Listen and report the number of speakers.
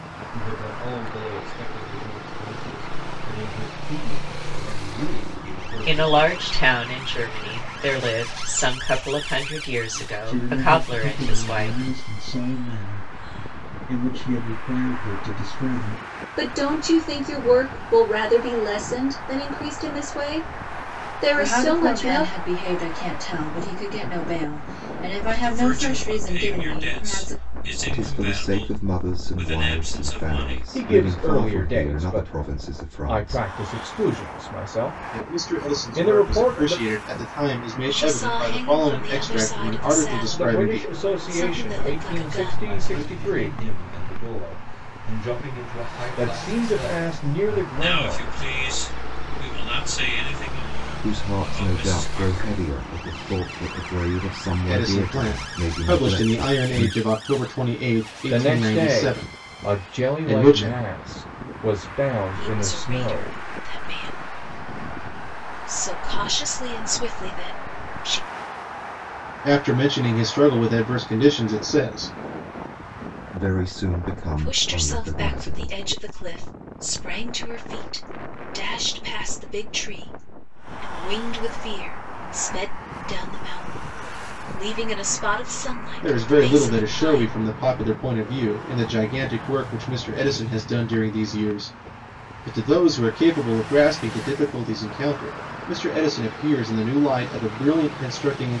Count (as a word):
ten